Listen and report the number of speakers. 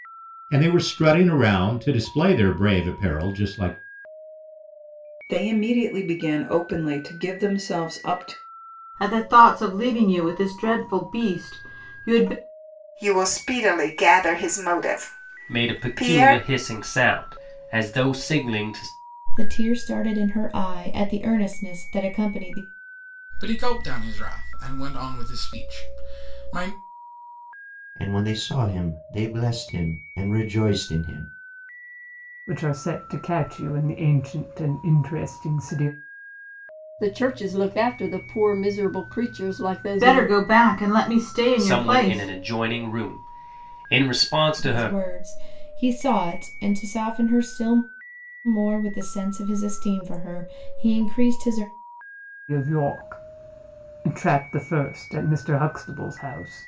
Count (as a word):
ten